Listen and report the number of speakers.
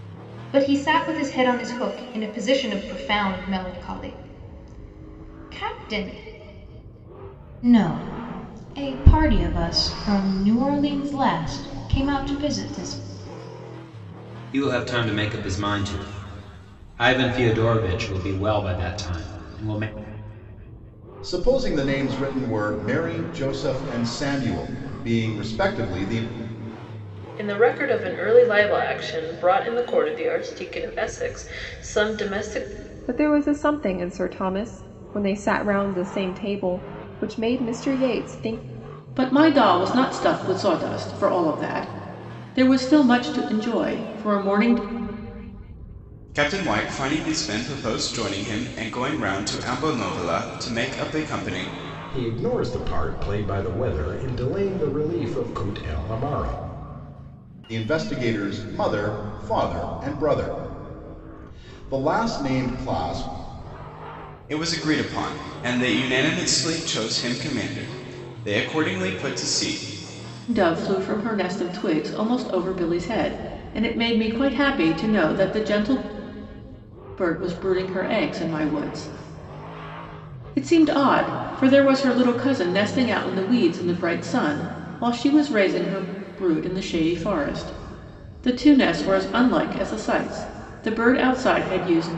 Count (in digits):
9